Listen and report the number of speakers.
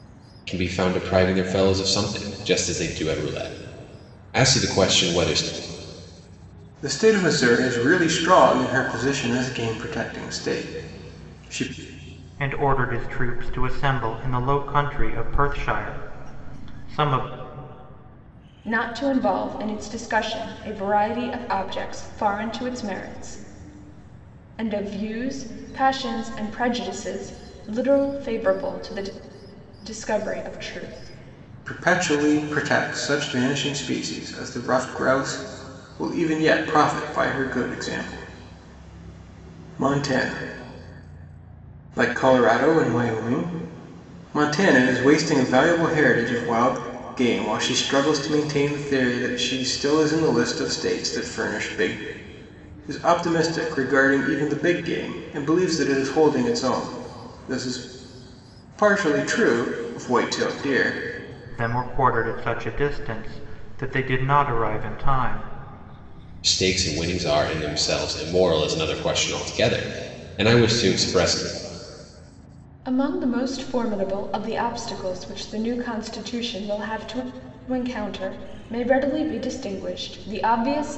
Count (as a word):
four